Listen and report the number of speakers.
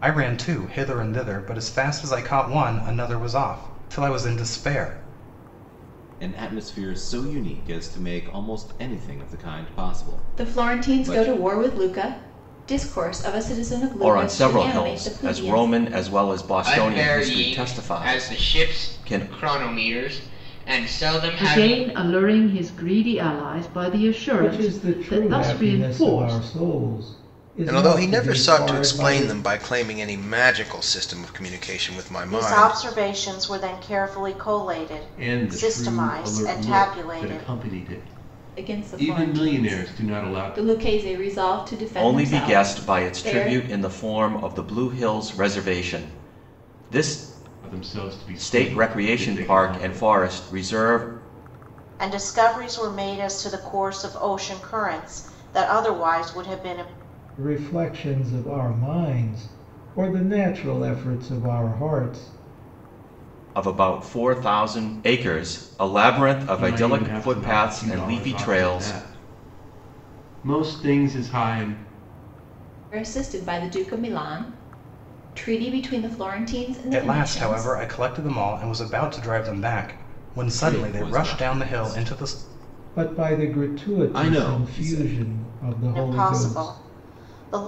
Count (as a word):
ten